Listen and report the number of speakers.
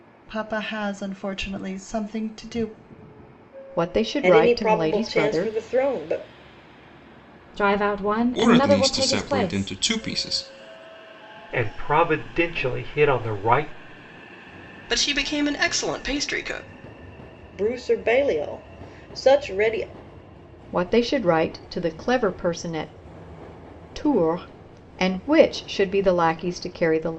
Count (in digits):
7